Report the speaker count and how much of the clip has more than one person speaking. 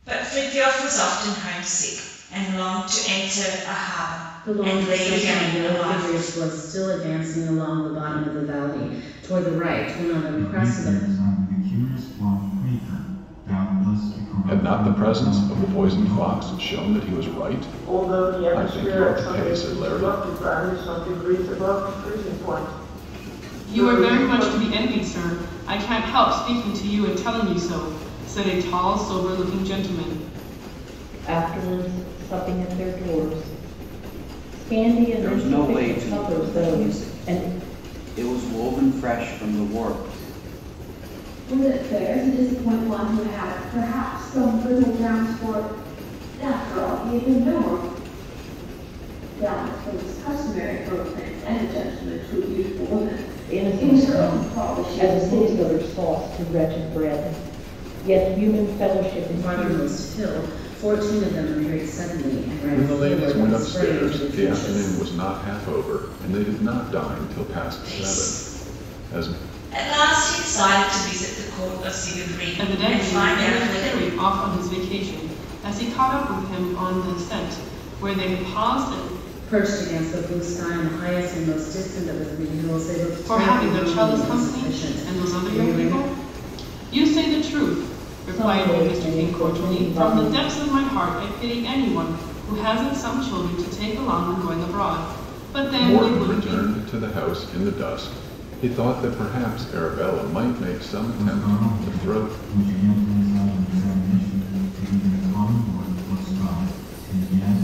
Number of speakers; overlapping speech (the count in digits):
9, about 24%